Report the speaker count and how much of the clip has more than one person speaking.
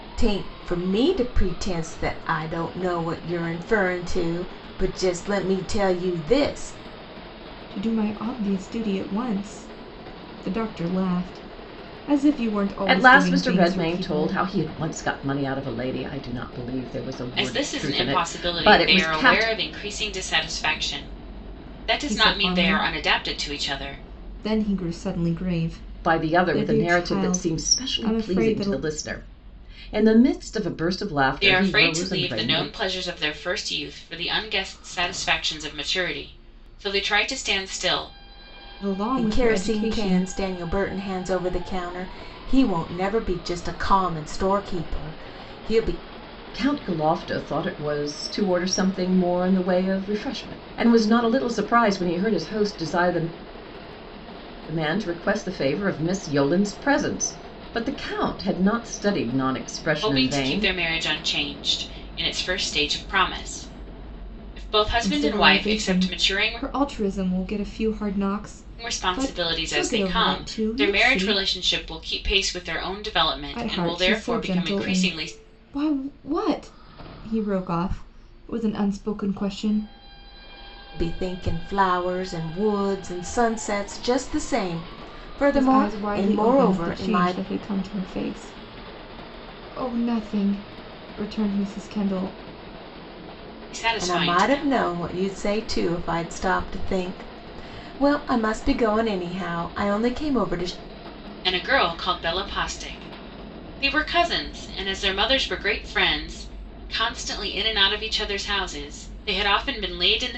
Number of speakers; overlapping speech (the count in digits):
4, about 19%